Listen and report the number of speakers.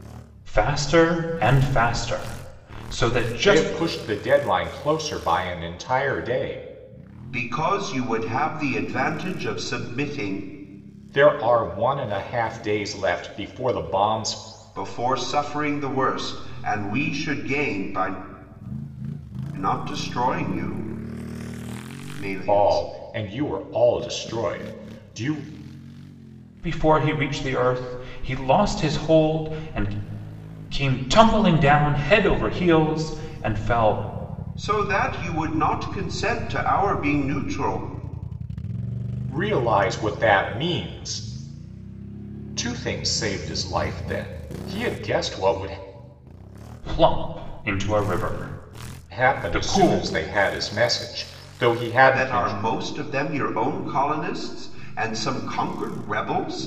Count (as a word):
three